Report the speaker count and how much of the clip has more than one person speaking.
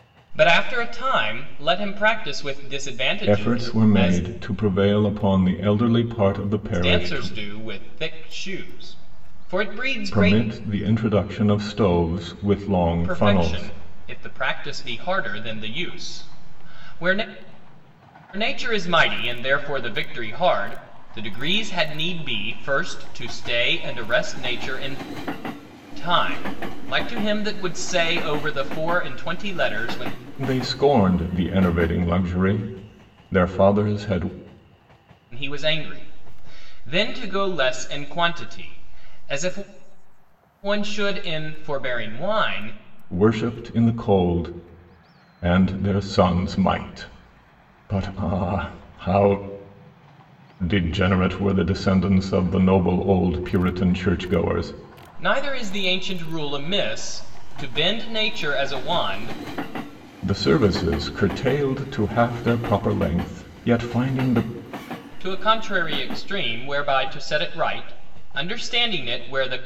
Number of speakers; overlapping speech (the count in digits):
2, about 4%